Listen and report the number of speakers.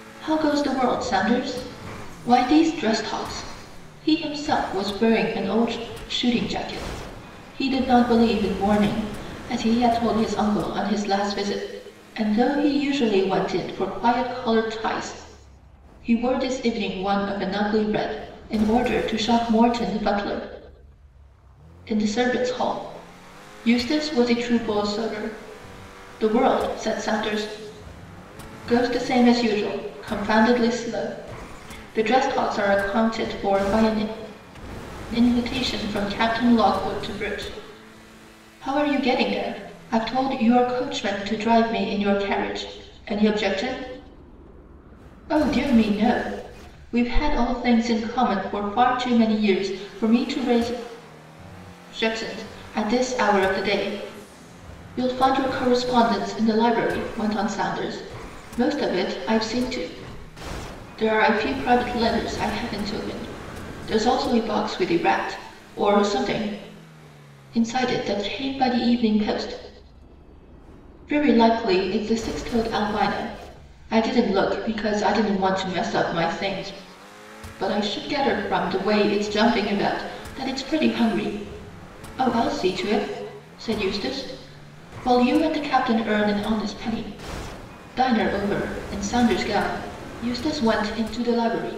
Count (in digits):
1